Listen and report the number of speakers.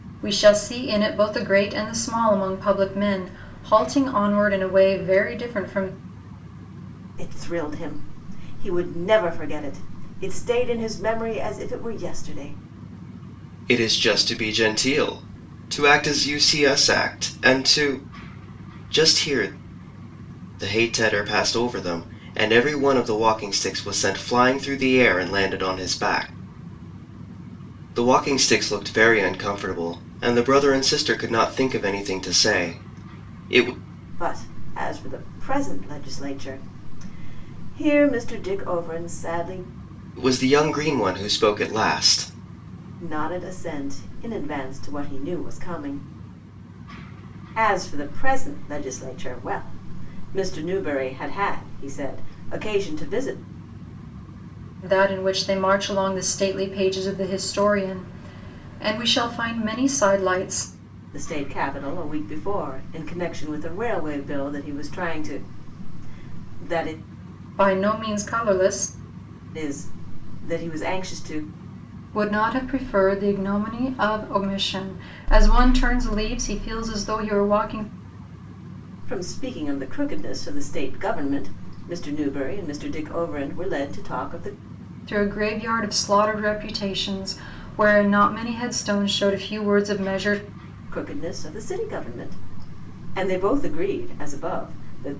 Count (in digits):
3